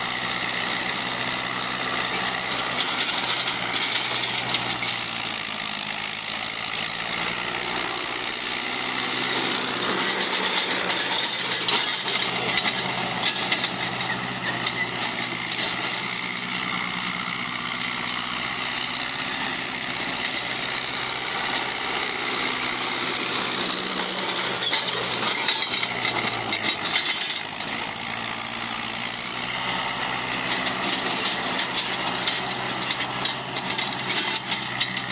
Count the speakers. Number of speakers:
0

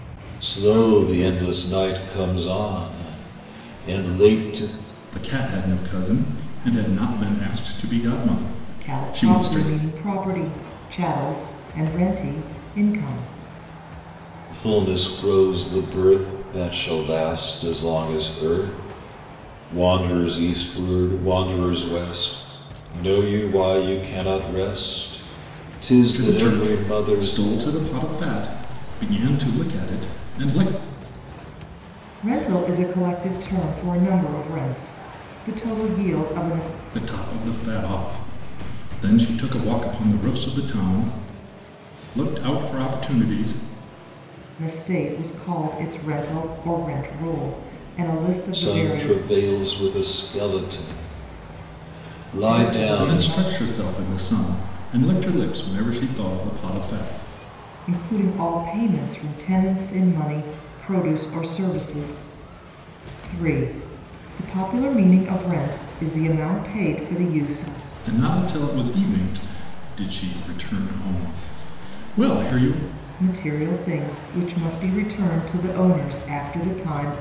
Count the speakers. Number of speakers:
3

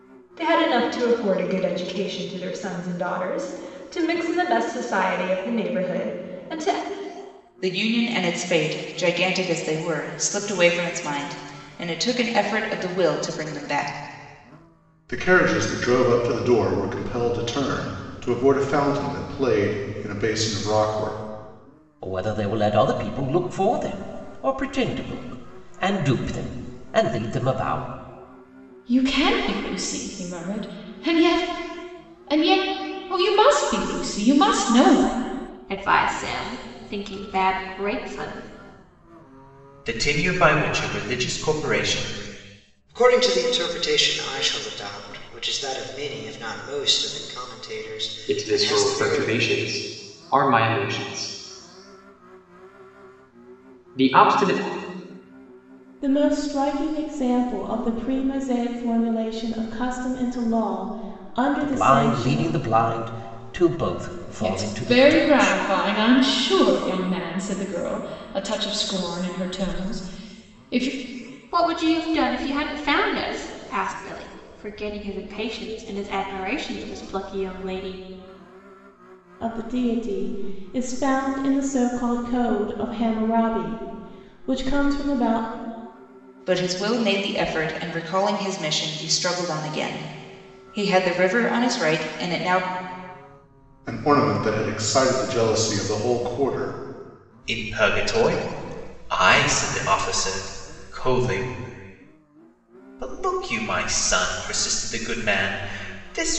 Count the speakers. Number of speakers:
10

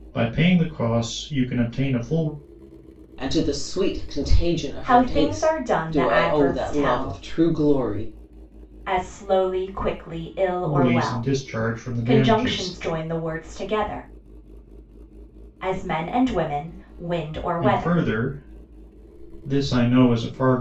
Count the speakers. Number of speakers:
3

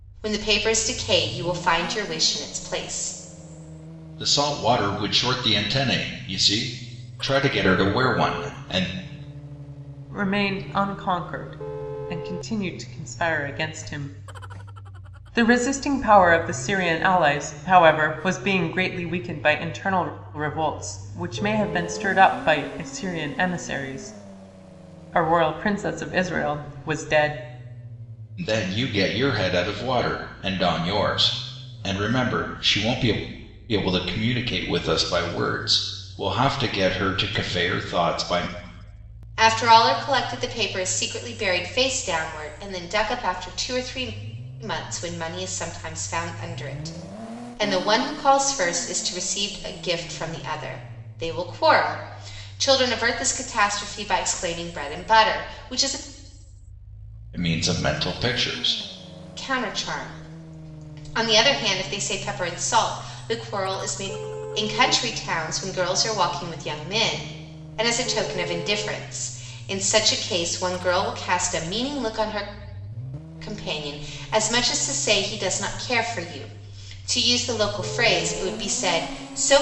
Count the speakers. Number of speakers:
3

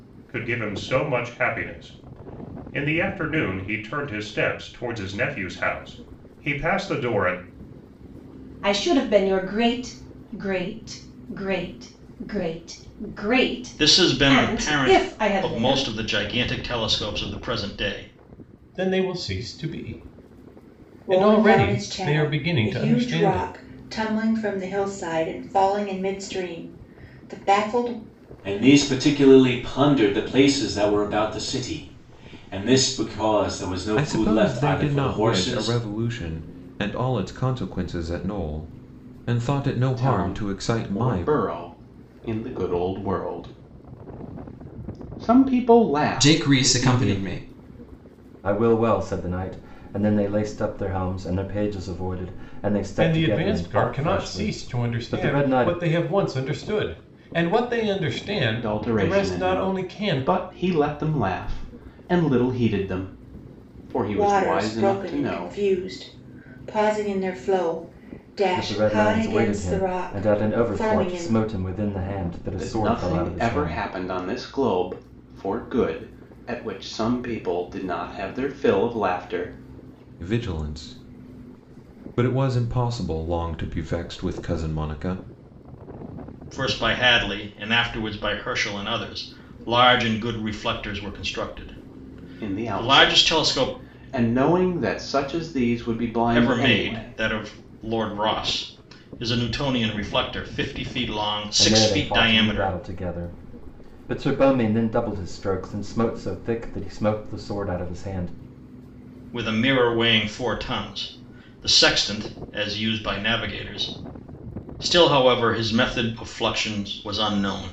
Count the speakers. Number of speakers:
10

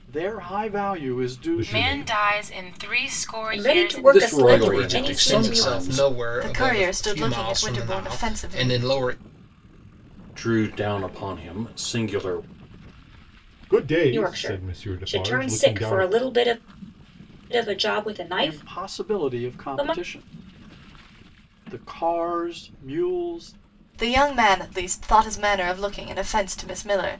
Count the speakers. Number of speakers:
7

